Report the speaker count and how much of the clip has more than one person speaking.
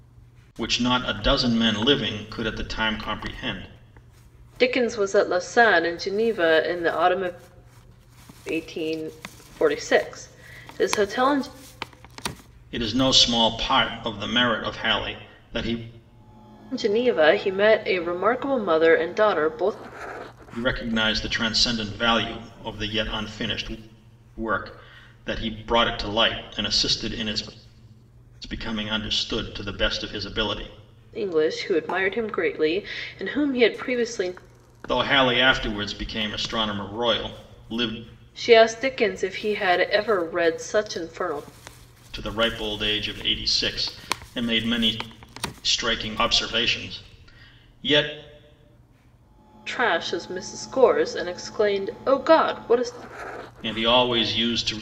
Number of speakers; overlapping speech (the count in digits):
2, no overlap